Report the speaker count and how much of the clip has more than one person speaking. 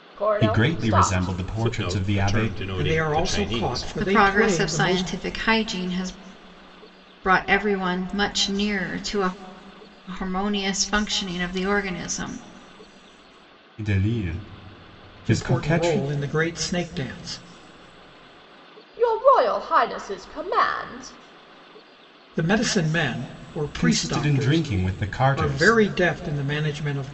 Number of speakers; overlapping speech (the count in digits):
5, about 24%